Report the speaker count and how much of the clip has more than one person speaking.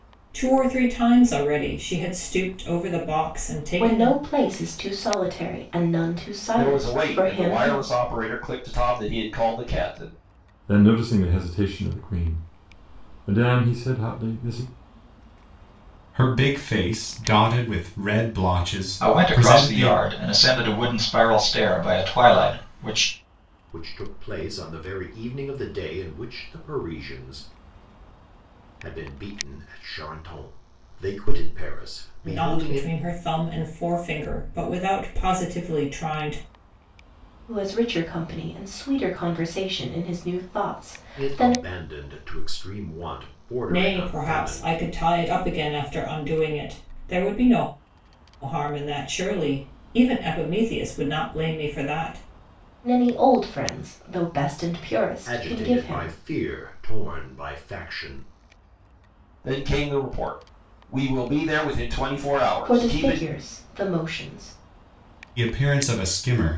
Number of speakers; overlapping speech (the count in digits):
7, about 9%